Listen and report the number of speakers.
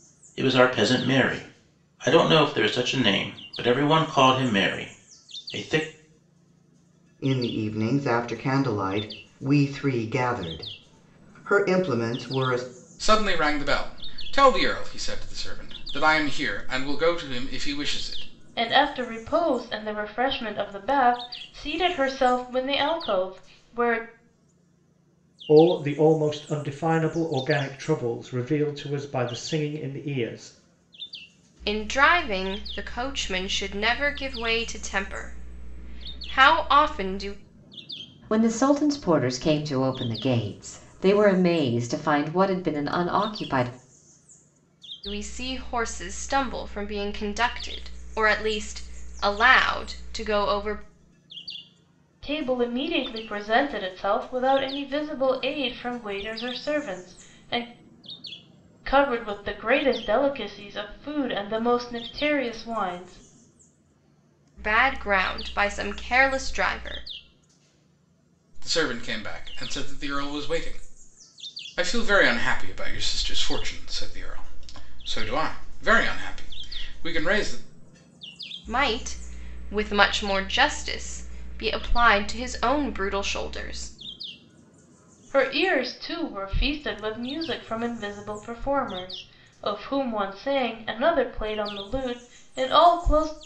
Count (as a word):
seven